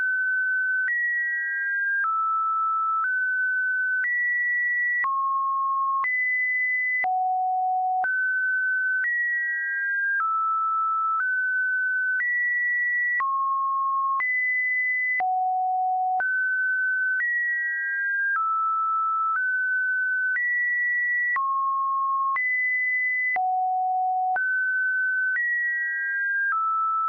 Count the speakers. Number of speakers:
0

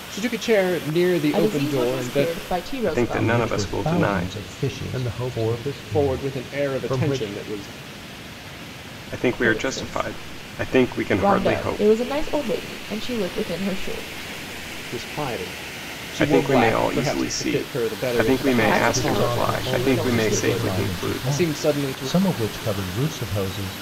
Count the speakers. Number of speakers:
5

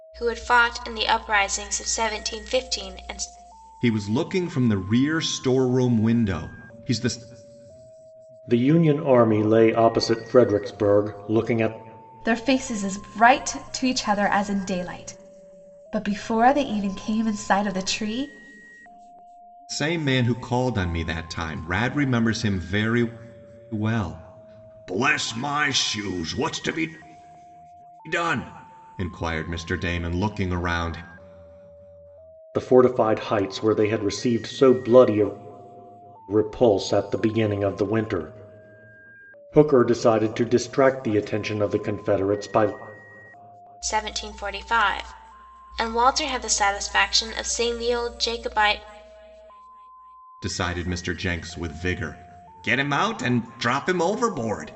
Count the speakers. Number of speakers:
4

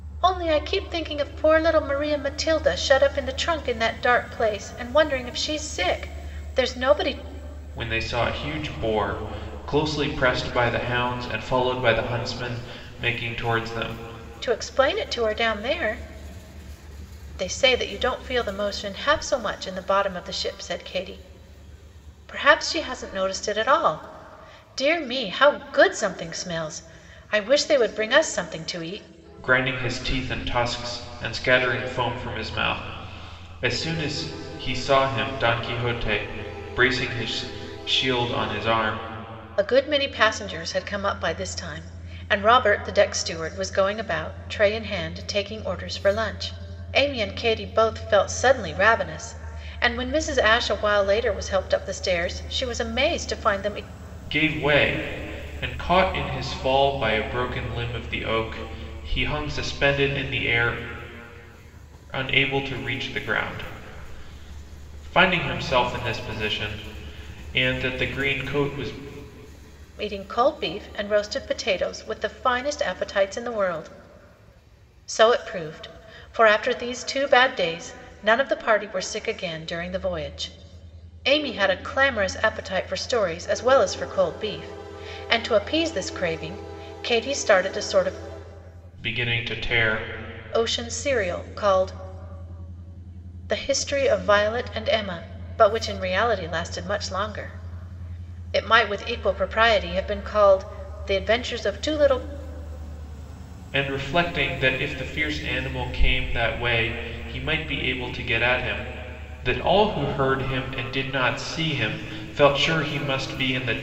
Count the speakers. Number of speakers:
2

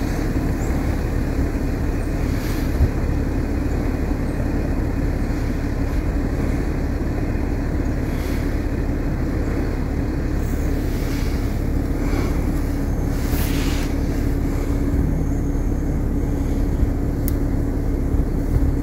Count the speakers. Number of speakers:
0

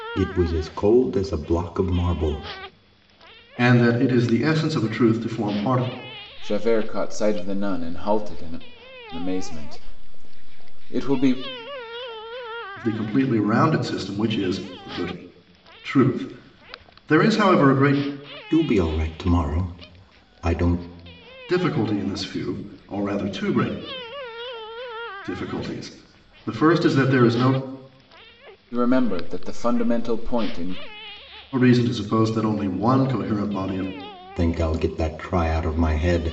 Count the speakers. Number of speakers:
3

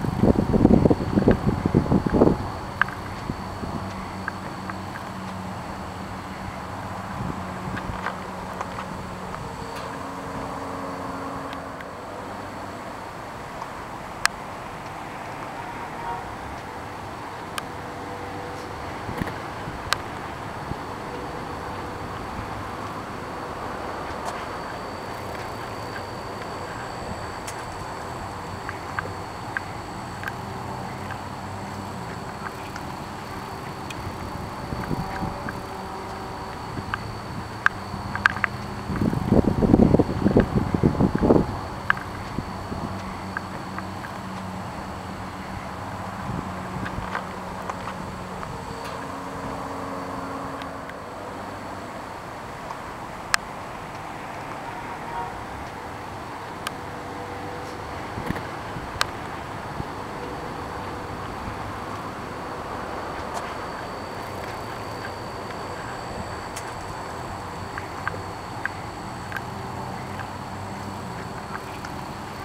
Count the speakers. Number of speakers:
0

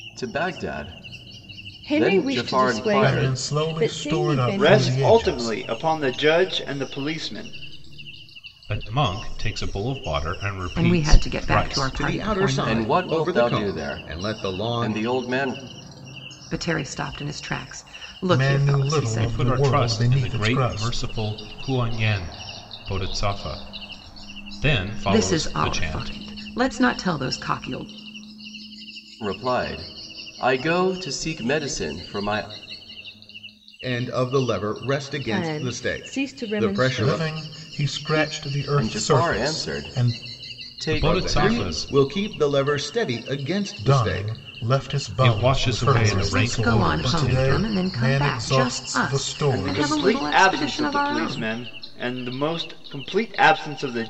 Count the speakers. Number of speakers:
7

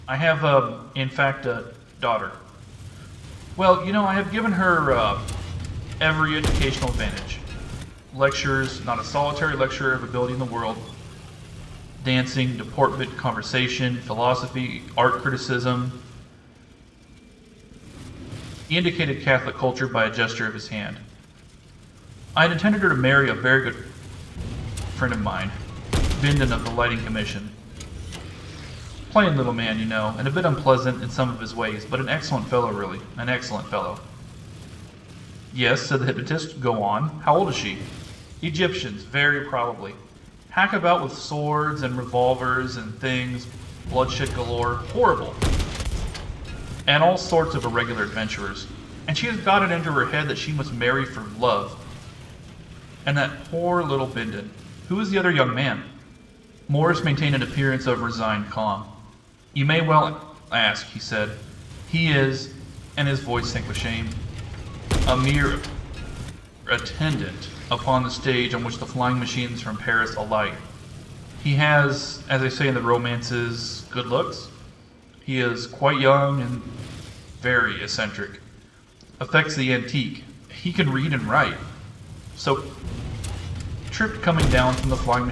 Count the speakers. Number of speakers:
1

